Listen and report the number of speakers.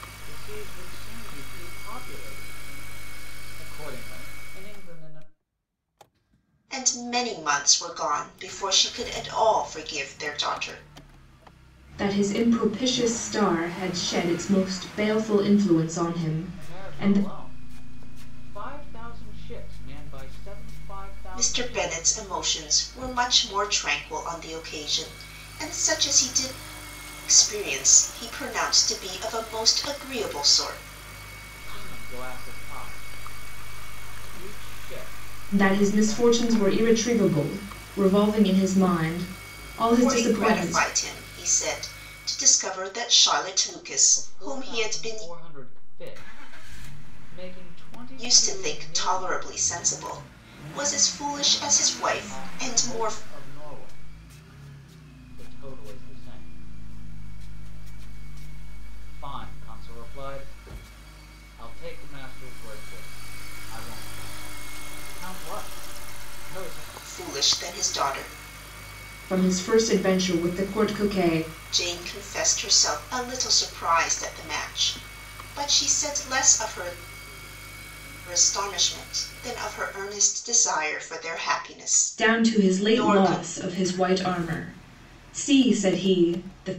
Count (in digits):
3